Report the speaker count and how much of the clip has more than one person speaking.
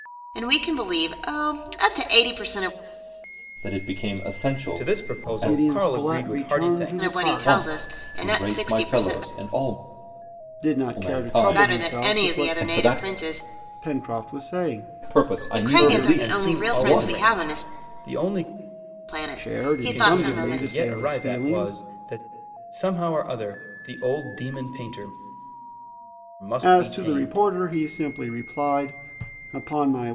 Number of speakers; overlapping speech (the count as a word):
four, about 42%